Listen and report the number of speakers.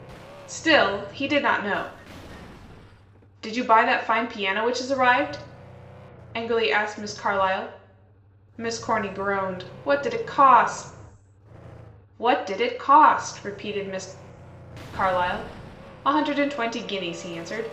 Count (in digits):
1